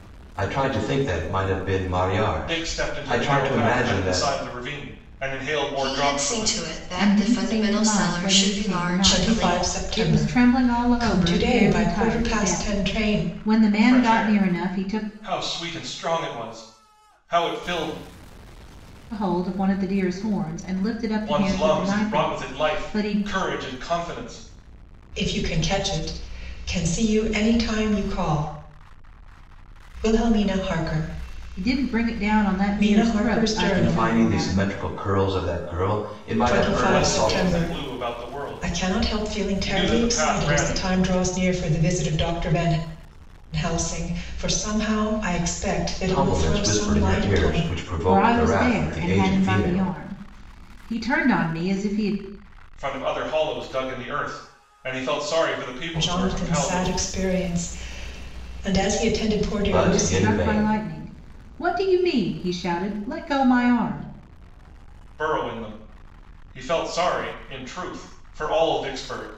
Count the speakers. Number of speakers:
five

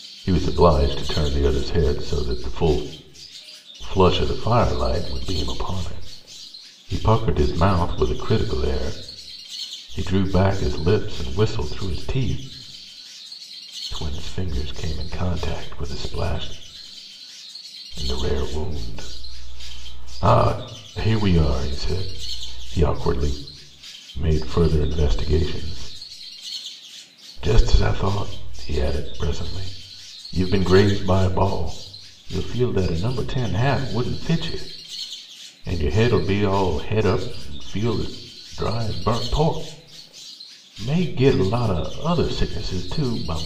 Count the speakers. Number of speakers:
one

